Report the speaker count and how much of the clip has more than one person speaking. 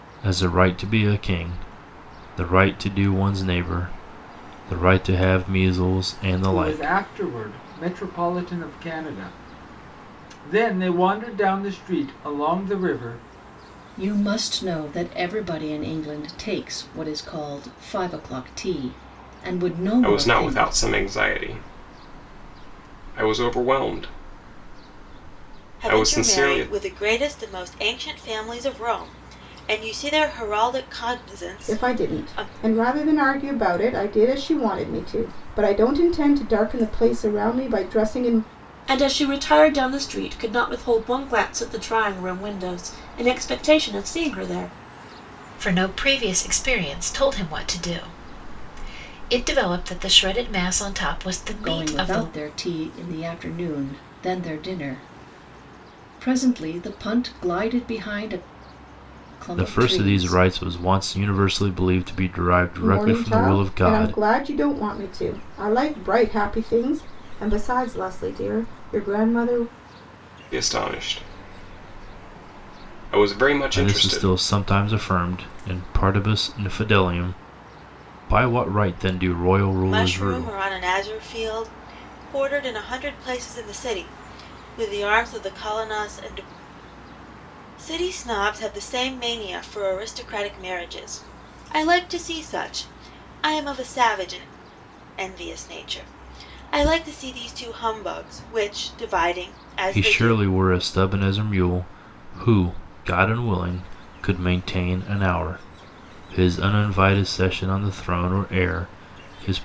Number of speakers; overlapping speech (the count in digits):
8, about 7%